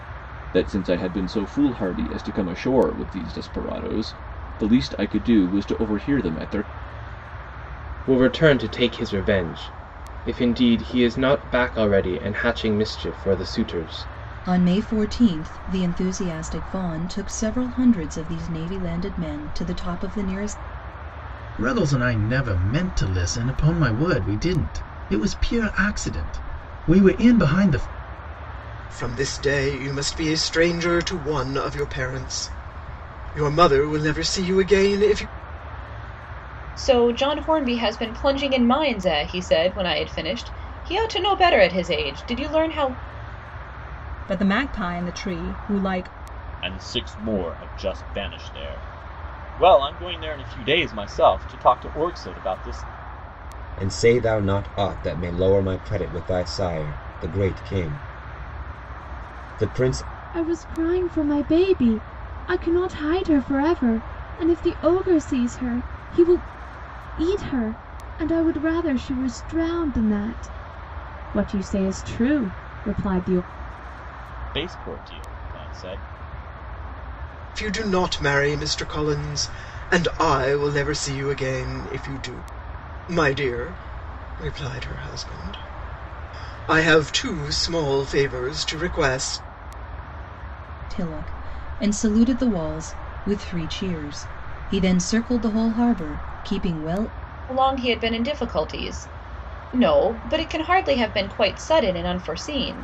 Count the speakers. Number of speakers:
10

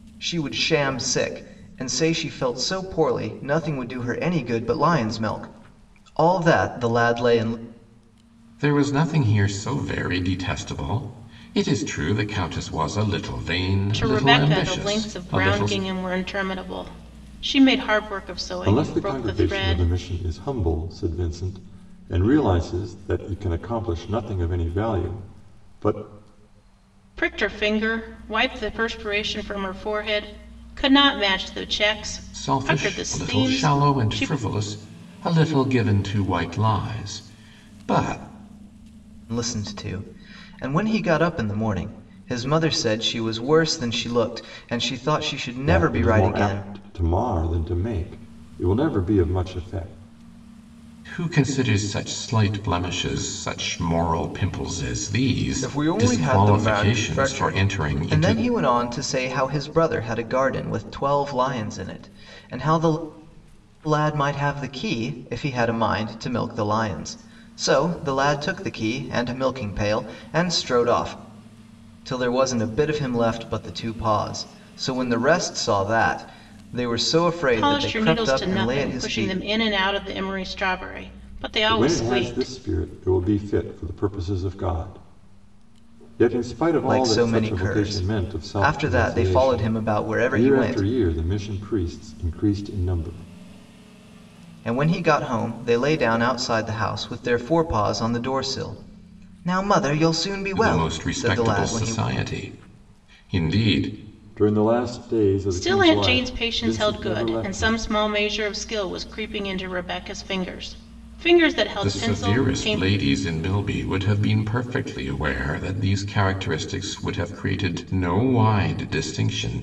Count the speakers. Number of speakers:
4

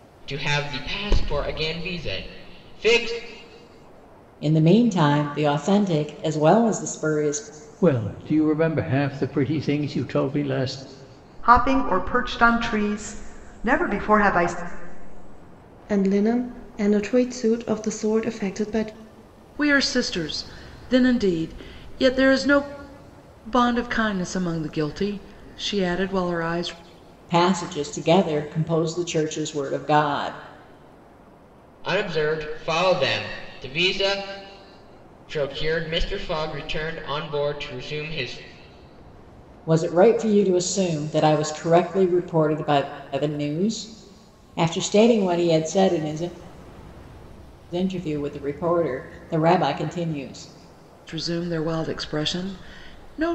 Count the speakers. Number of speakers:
6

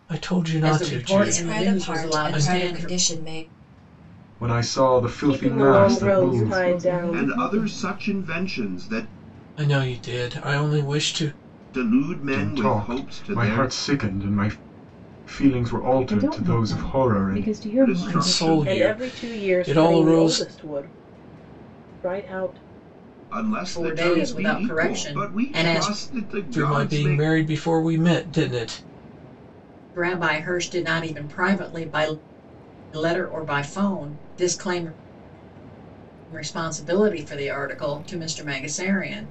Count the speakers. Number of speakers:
7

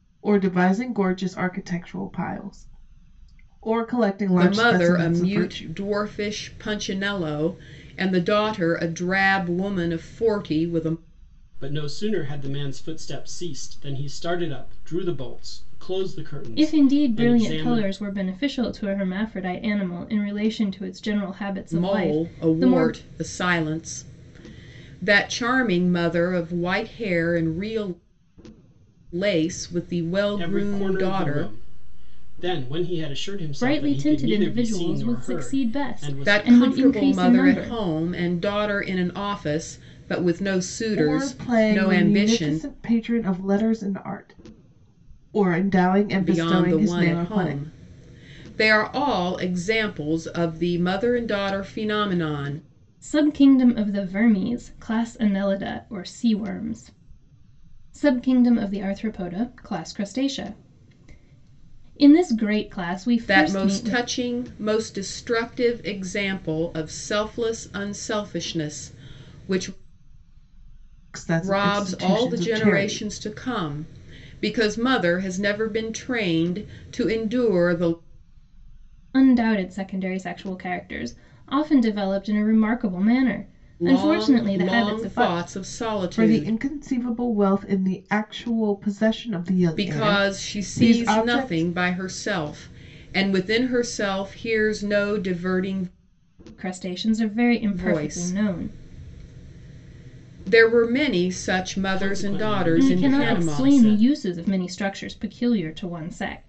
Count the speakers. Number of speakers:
4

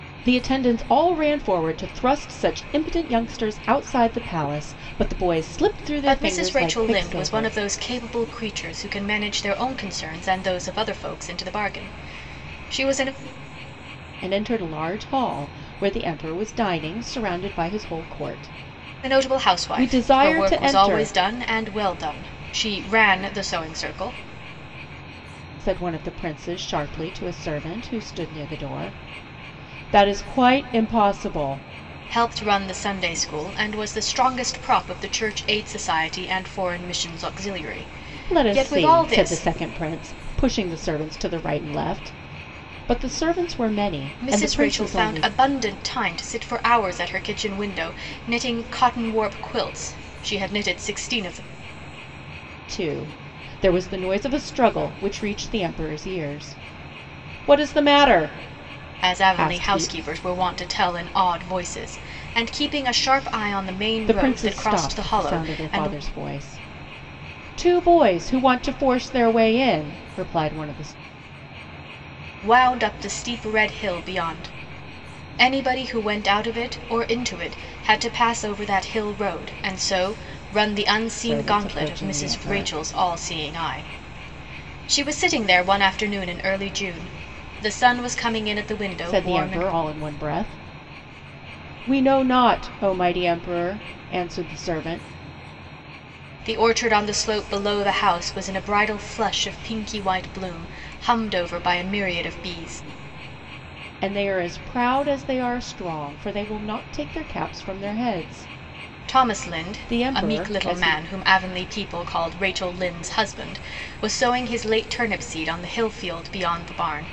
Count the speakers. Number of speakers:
2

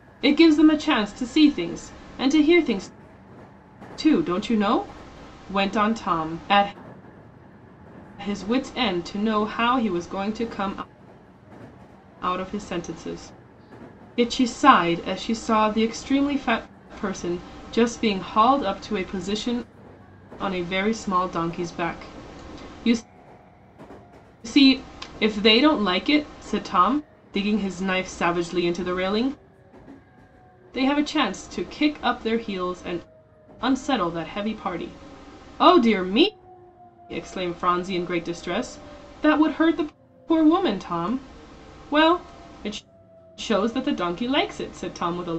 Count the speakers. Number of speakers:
1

